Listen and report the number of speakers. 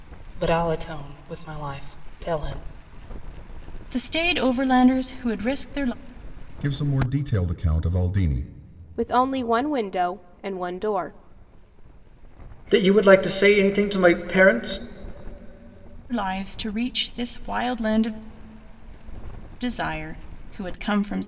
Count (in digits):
5